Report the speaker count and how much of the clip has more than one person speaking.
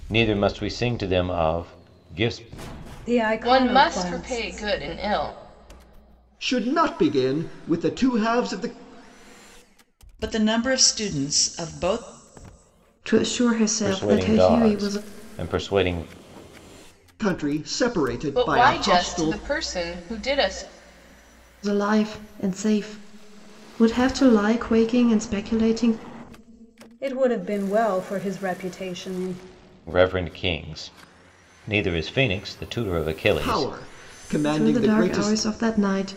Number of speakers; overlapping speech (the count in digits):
6, about 14%